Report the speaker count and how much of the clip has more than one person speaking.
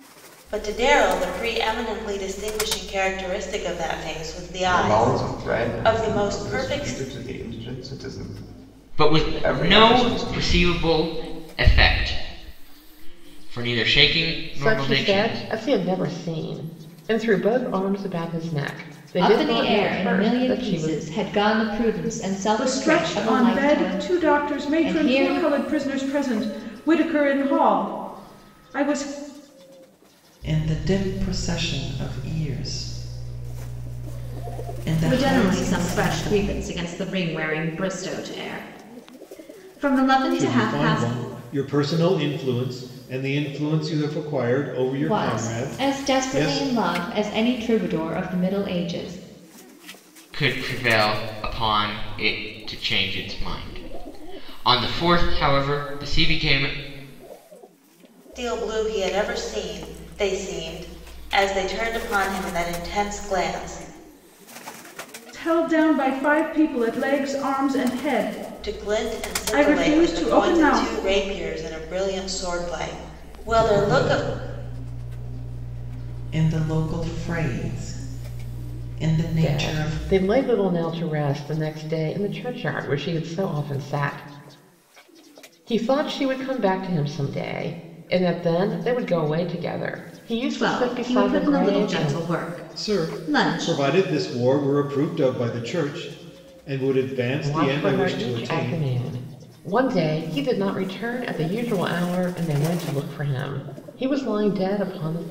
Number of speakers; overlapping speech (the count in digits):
9, about 21%